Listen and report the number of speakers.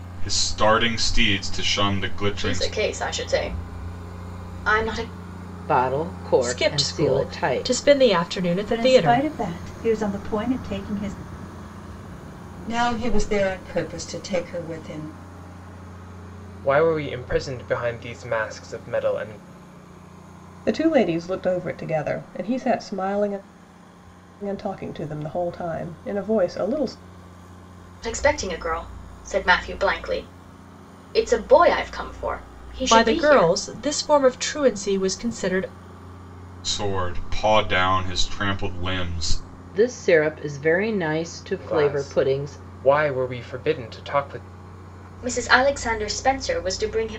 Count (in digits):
8